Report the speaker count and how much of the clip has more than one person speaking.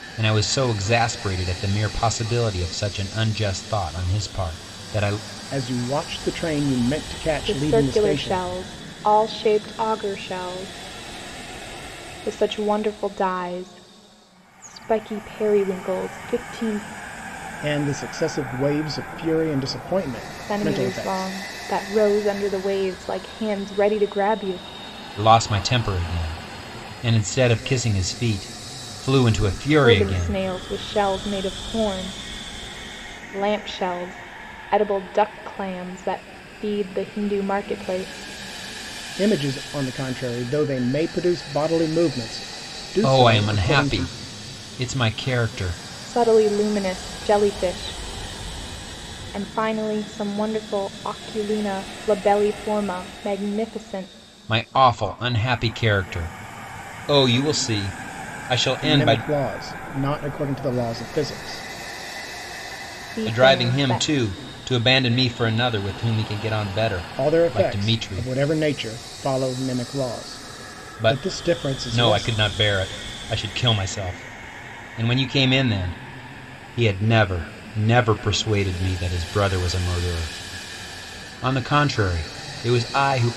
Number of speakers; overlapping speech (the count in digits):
3, about 9%